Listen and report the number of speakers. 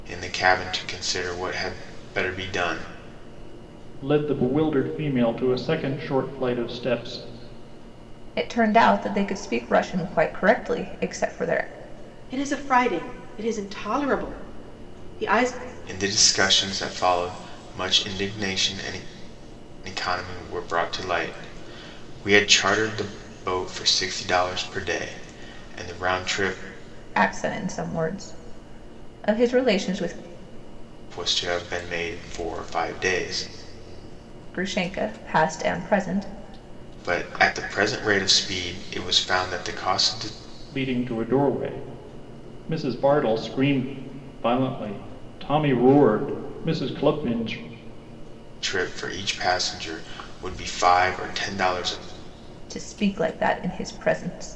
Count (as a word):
four